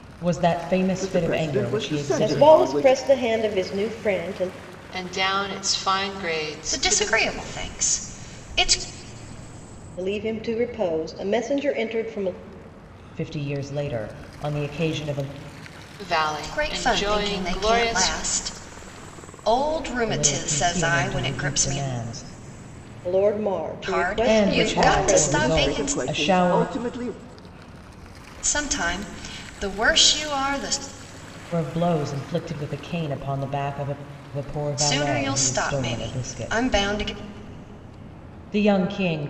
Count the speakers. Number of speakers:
5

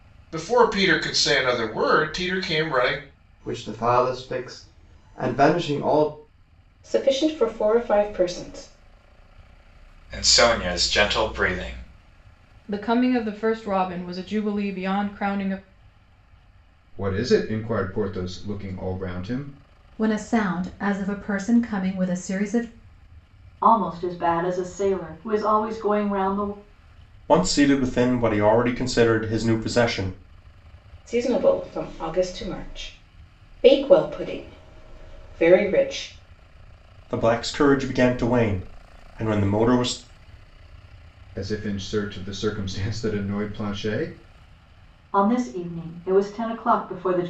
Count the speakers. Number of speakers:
9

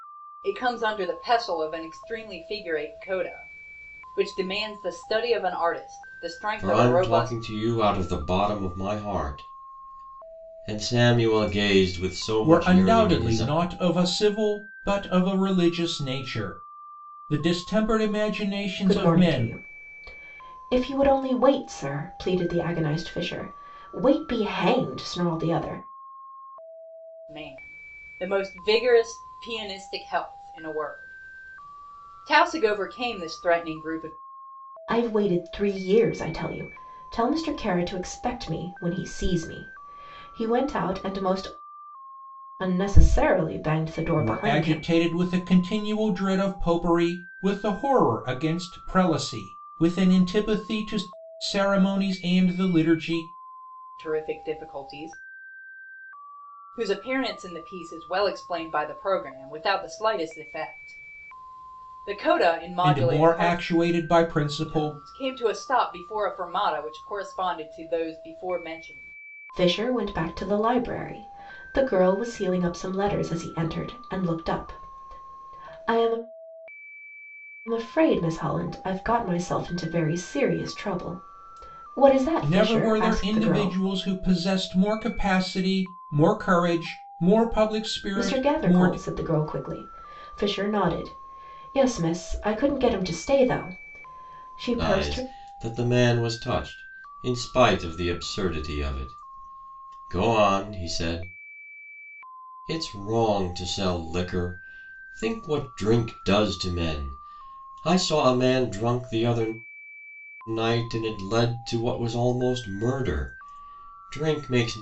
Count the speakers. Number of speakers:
4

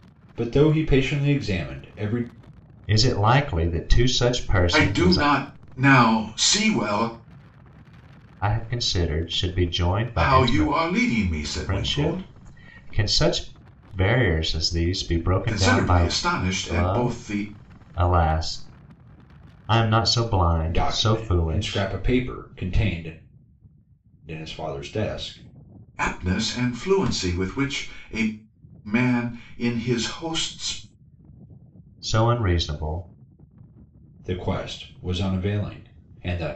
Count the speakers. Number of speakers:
3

